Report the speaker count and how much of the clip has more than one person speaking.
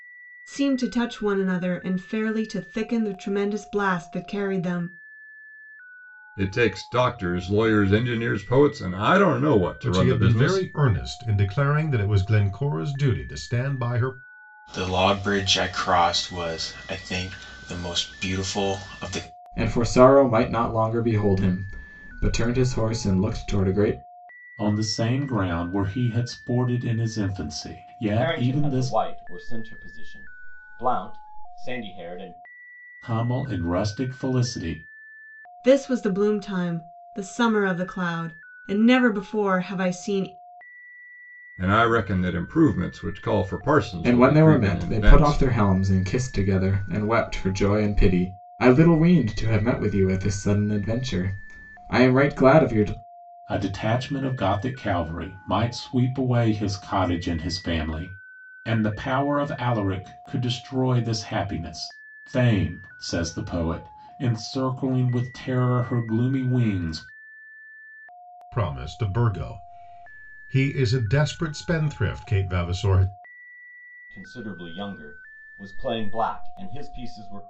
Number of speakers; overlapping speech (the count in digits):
7, about 4%